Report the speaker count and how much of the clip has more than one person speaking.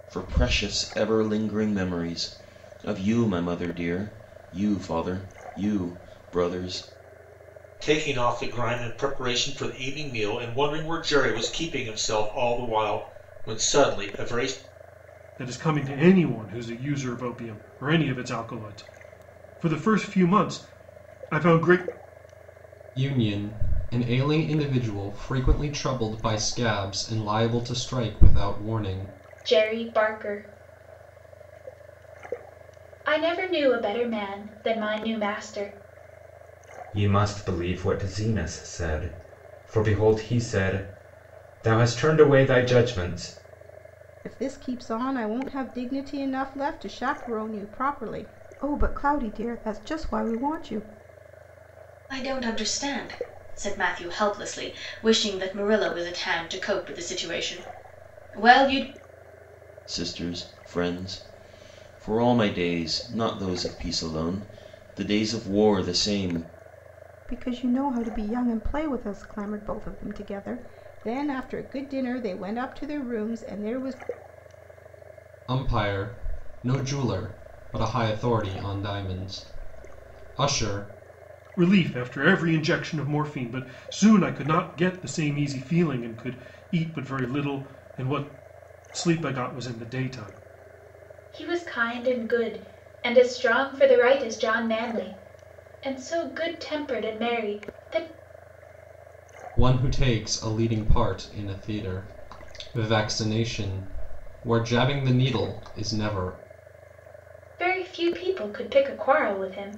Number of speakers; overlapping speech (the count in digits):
8, no overlap